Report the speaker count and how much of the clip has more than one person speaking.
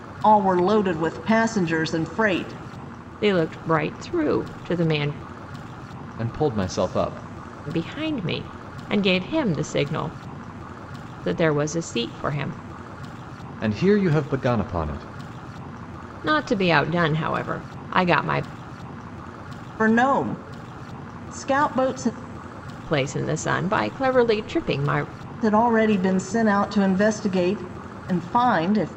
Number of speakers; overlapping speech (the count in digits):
3, no overlap